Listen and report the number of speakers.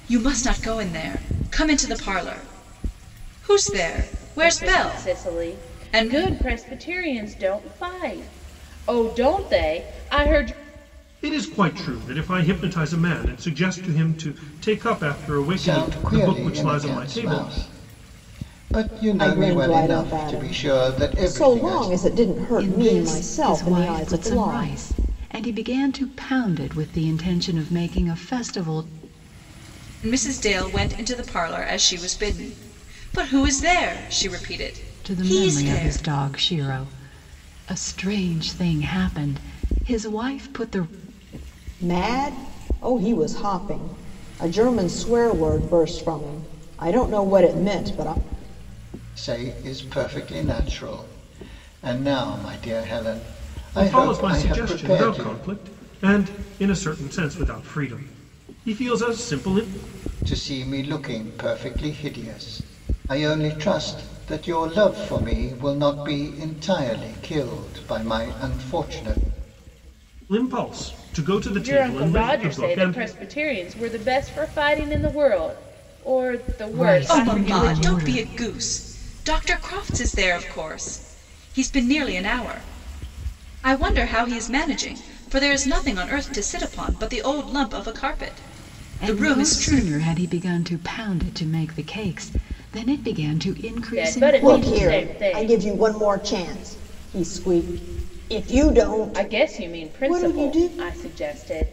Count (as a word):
six